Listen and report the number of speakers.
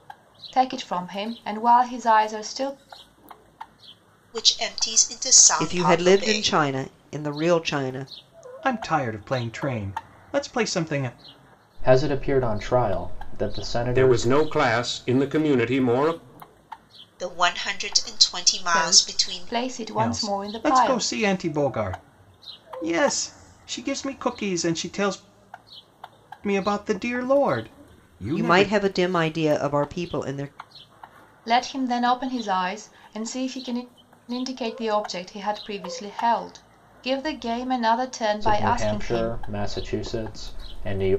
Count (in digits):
6